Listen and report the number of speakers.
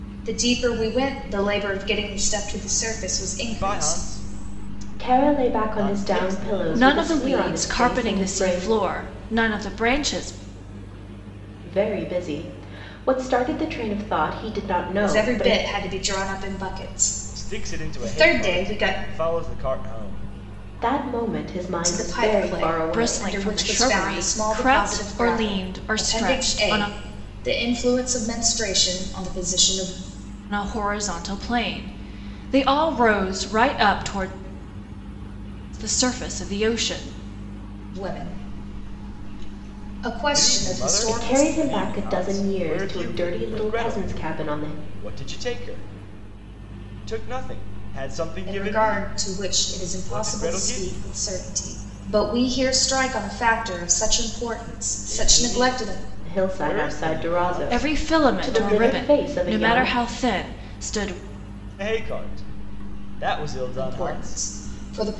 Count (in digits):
4